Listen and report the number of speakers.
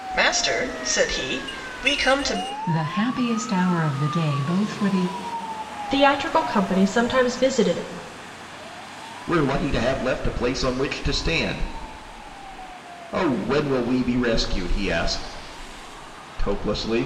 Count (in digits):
4